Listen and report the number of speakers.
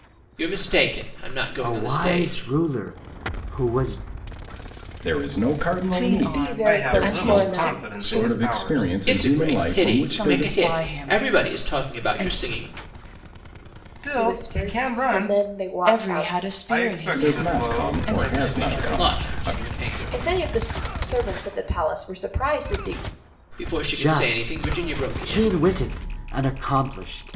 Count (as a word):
six